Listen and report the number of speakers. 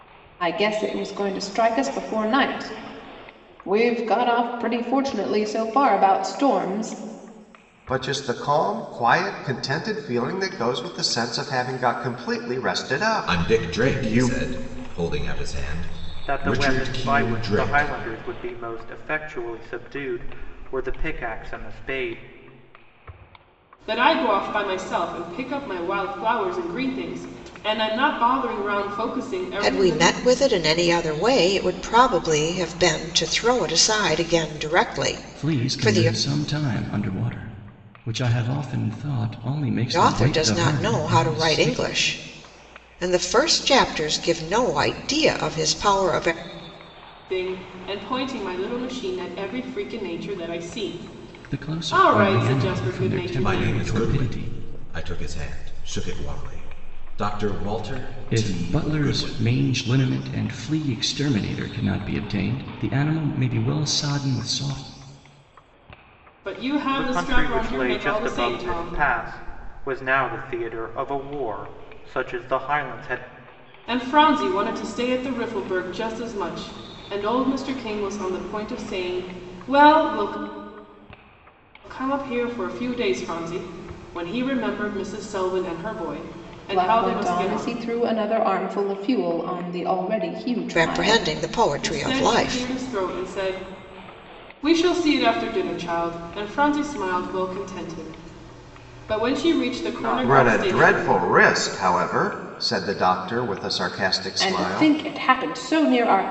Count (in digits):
7